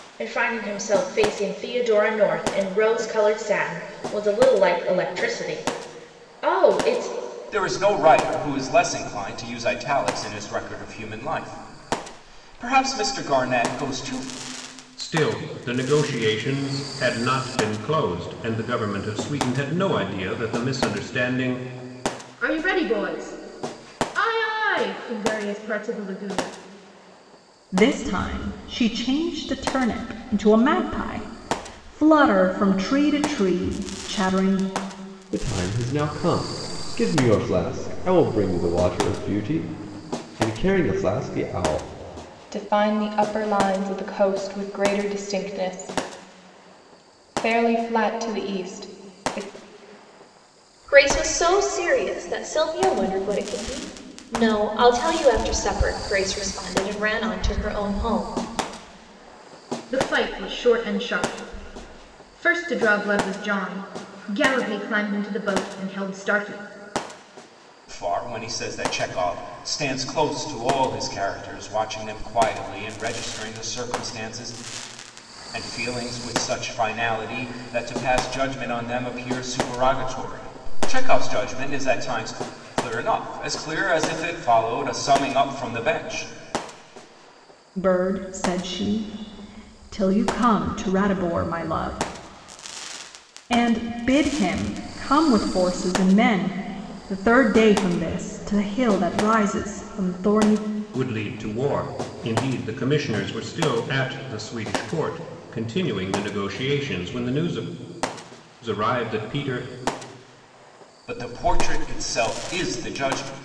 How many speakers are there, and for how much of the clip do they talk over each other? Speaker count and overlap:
8, no overlap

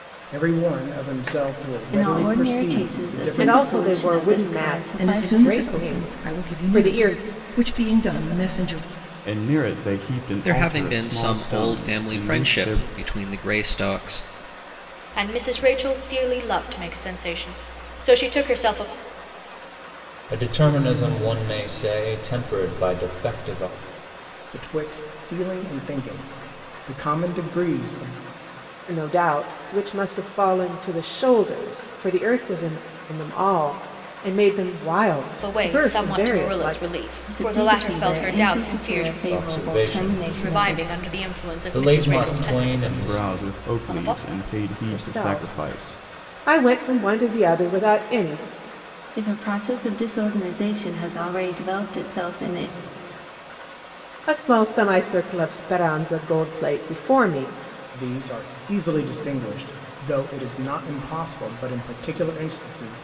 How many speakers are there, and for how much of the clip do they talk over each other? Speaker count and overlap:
8, about 27%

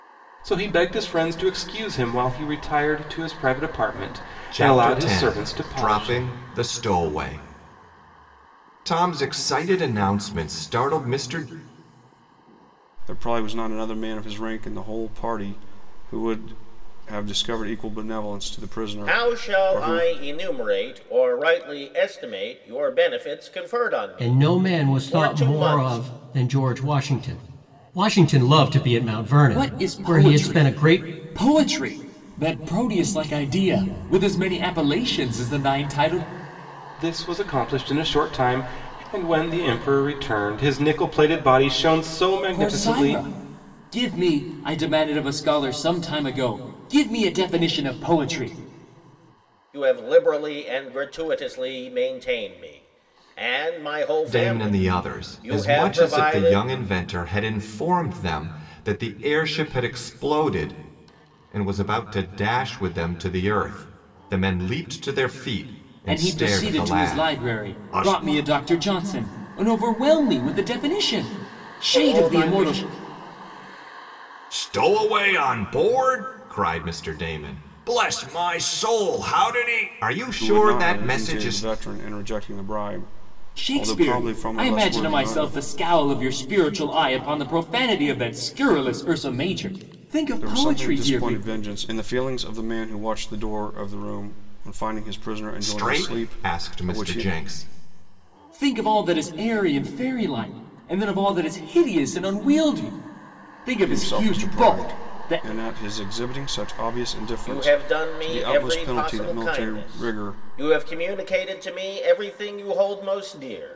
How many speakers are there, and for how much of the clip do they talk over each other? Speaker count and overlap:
6, about 21%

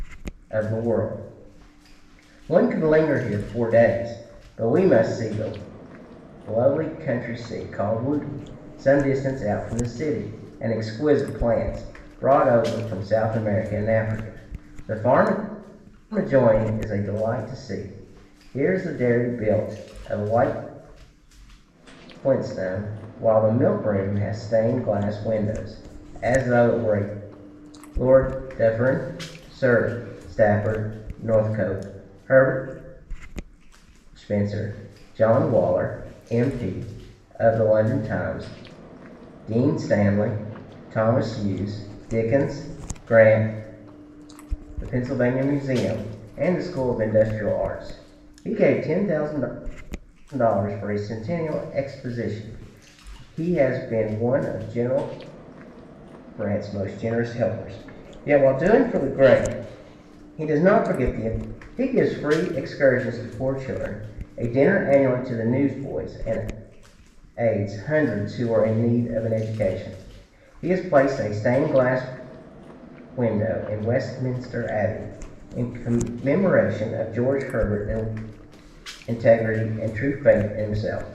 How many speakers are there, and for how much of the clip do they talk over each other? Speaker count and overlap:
1, no overlap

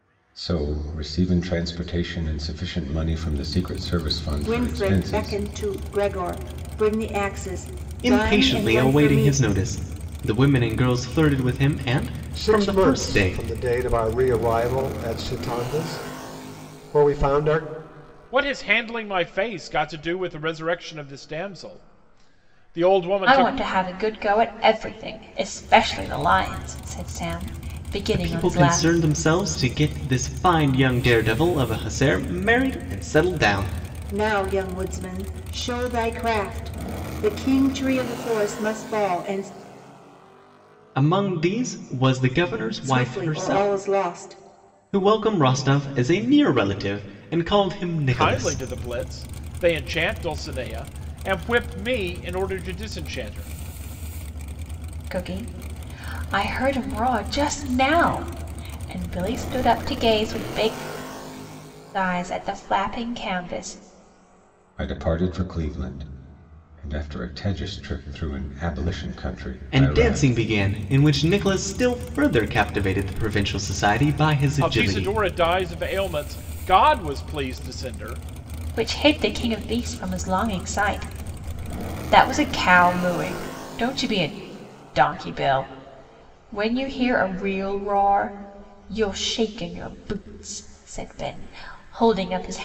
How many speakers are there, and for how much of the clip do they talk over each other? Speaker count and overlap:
6, about 8%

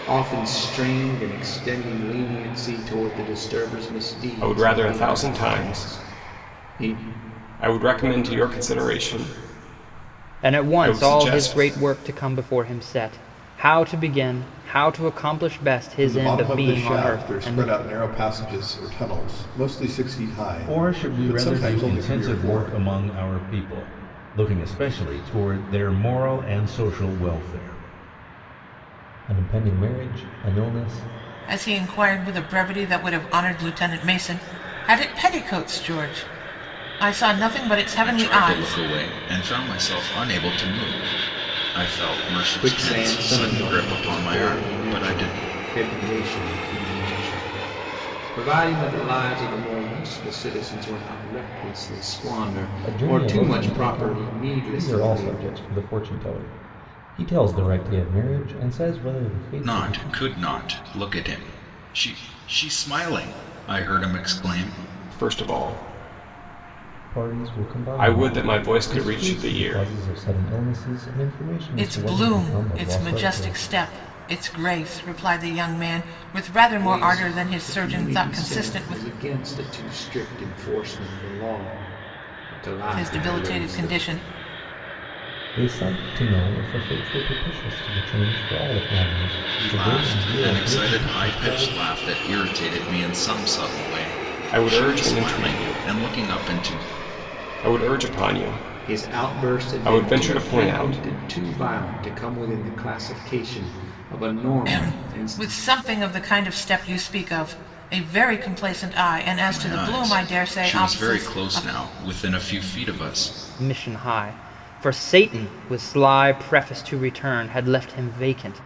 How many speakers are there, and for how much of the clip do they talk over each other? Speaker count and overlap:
8, about 27%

